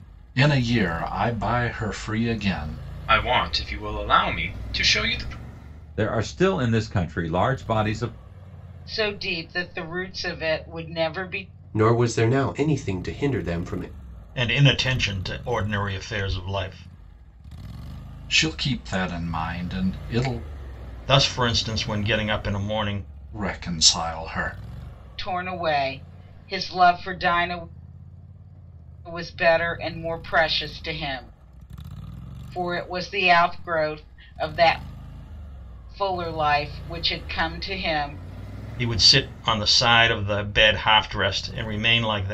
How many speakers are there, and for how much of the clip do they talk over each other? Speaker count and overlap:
six, no overlap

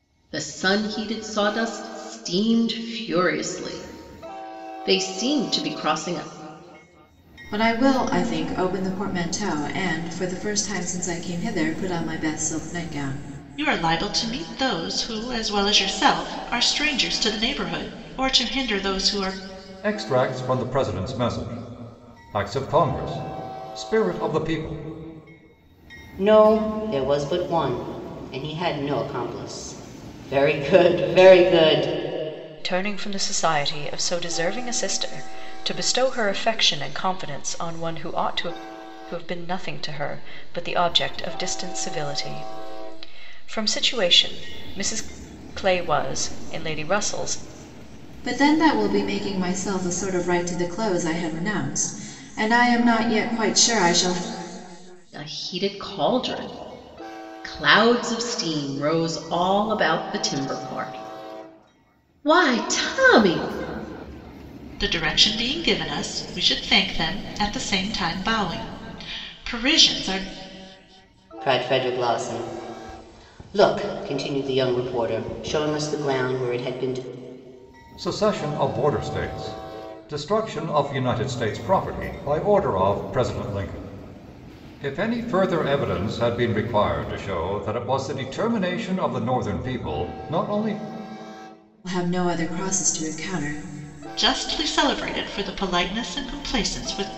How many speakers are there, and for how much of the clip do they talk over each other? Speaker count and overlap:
six, no overlap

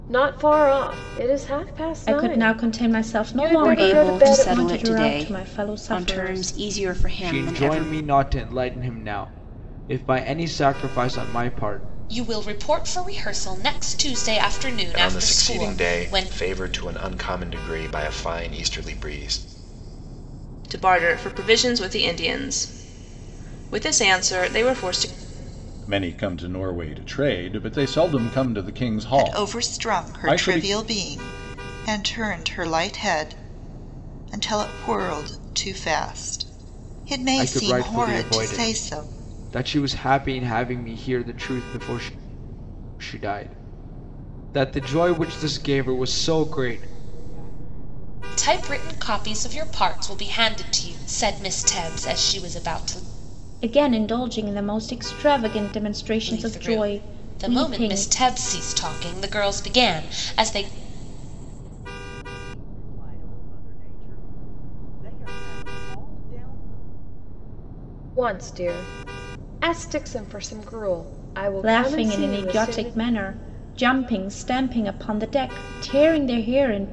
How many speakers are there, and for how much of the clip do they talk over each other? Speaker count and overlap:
ten, about 27%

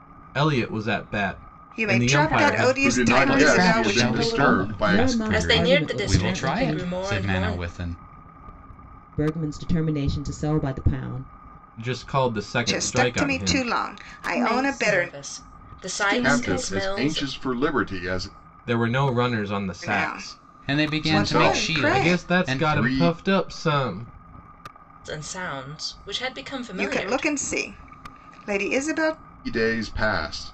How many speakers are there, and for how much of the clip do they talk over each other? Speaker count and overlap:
seven, about 44%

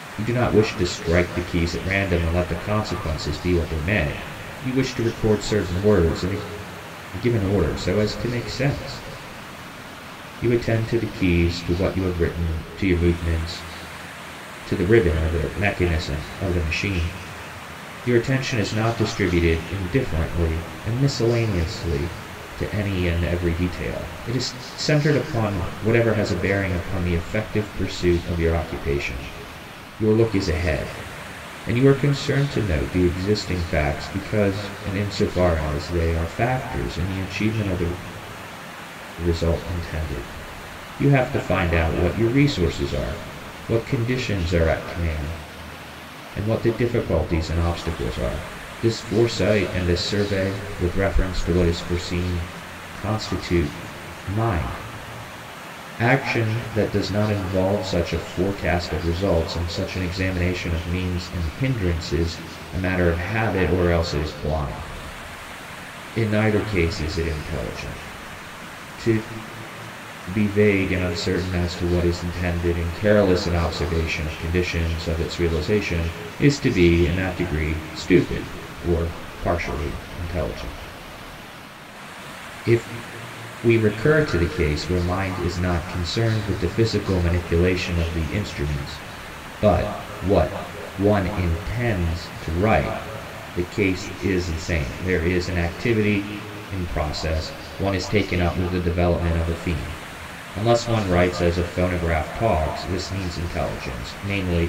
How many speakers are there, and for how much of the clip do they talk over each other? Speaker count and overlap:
one, no overlap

